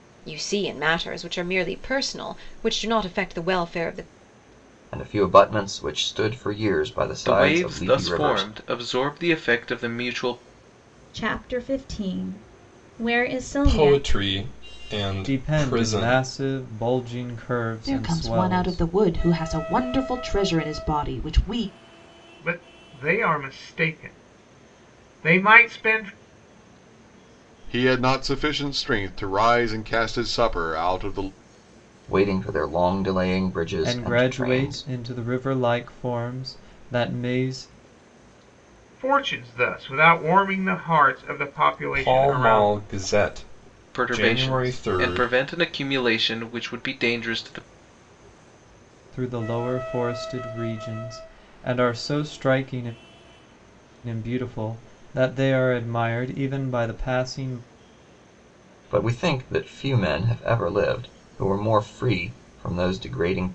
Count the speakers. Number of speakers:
nine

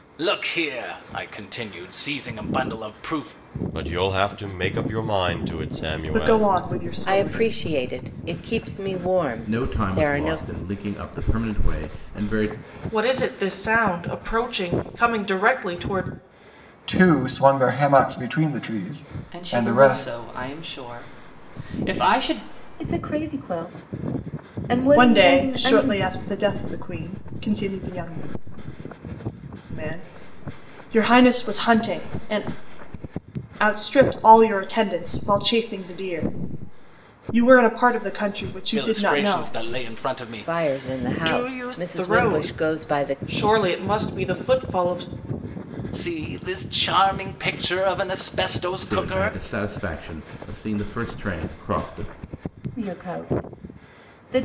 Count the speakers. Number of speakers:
nine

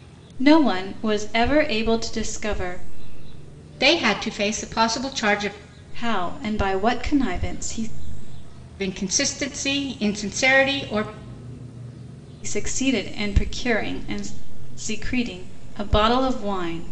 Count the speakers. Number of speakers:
two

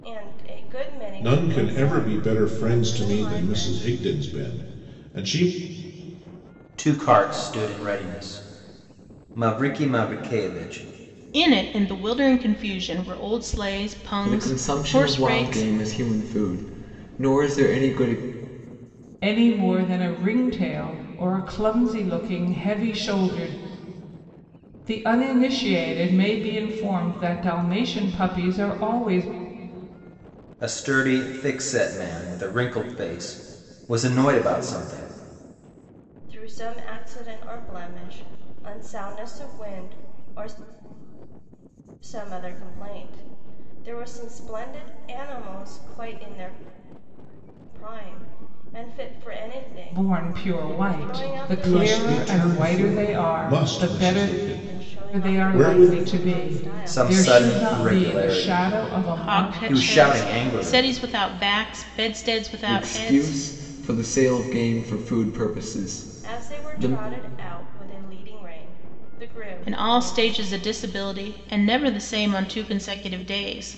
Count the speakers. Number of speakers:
six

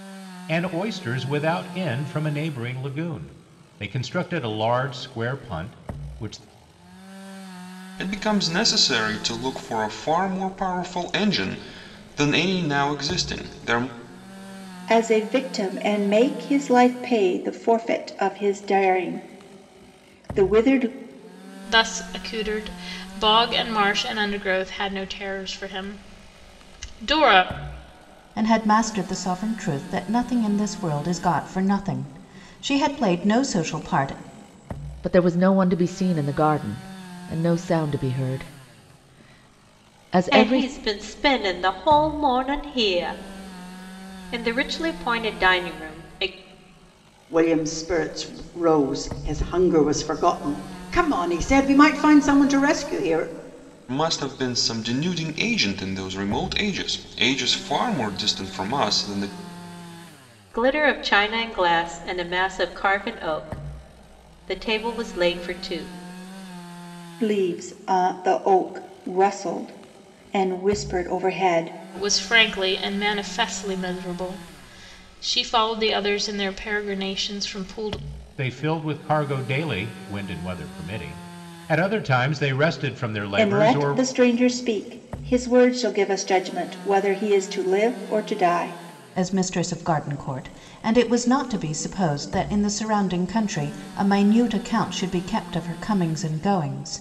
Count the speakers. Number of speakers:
eight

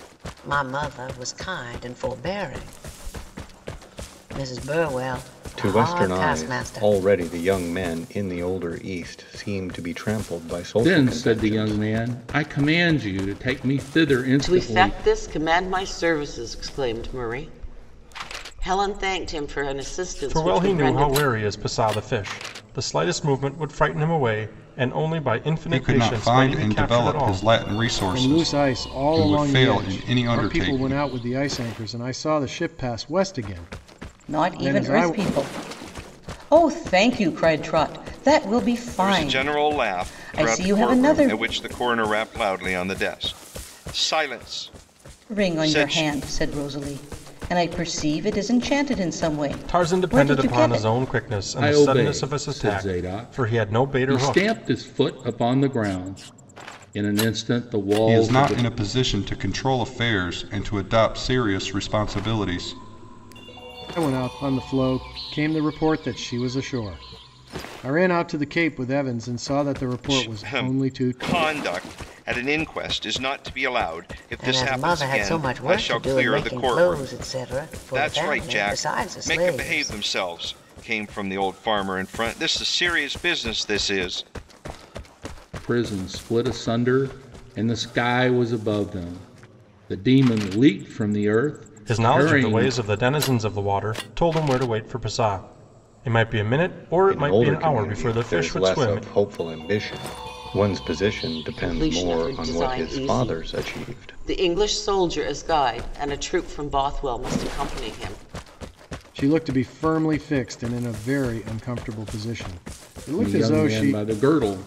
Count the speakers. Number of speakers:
nine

